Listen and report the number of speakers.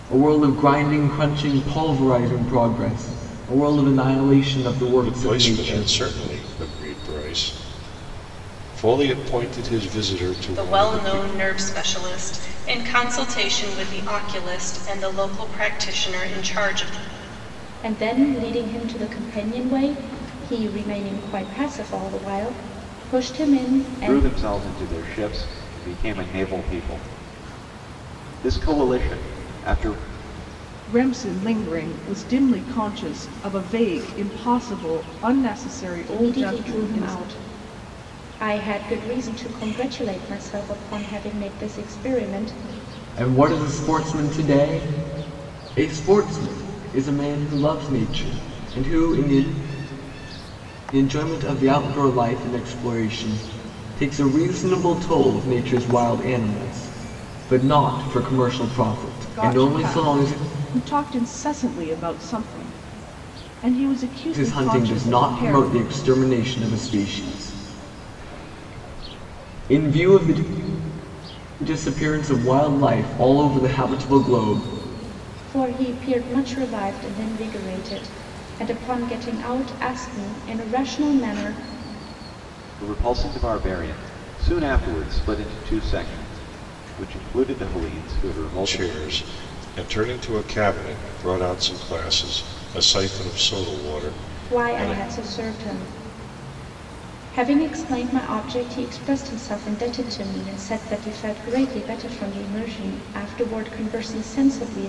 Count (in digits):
6